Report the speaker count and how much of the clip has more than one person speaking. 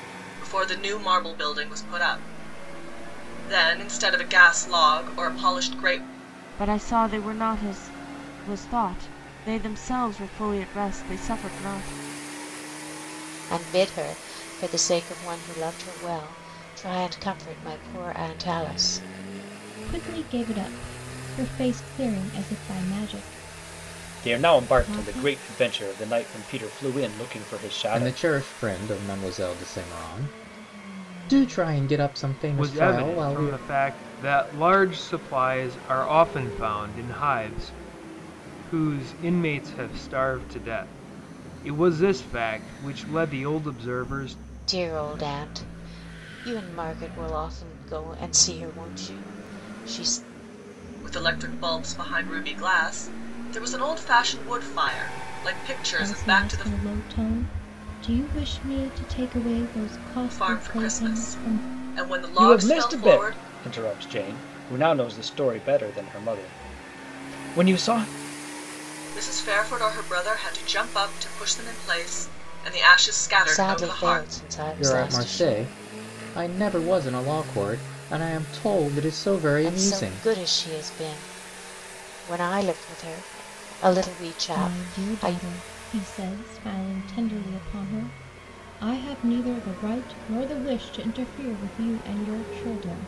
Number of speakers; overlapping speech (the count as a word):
seven, about 10%